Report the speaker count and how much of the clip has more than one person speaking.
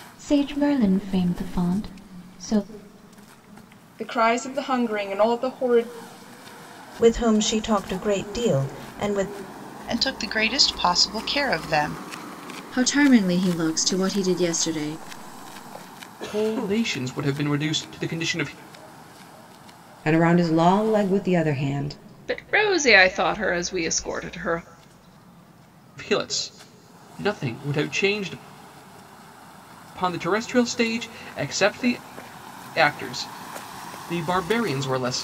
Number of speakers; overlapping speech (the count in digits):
8, no overlap